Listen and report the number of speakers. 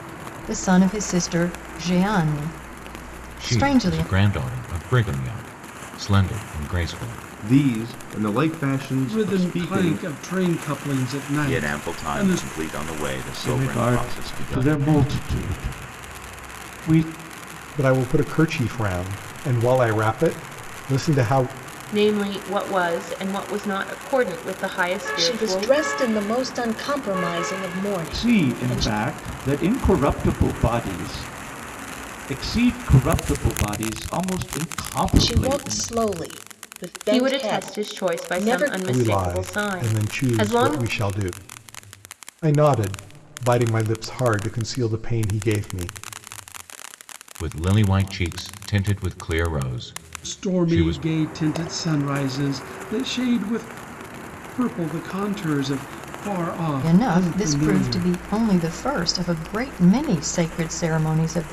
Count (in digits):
9